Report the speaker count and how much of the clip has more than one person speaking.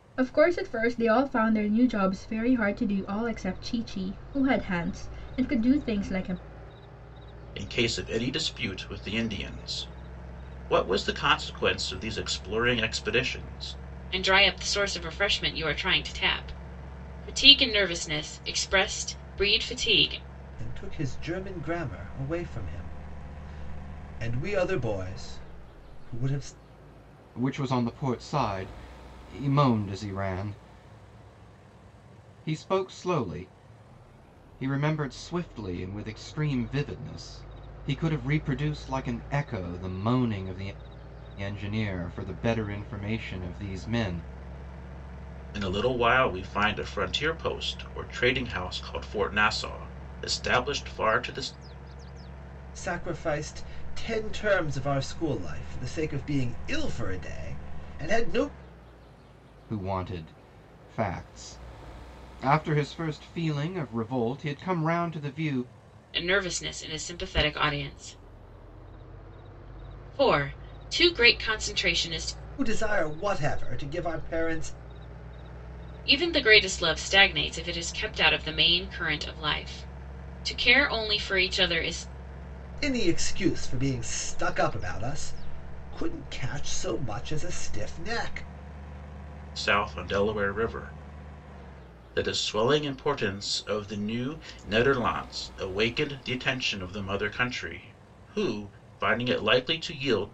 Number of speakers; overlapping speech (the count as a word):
five, no overlap